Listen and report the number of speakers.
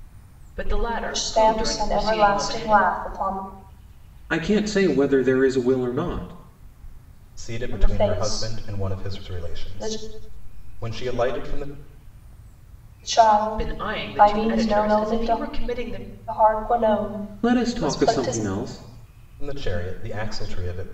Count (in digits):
4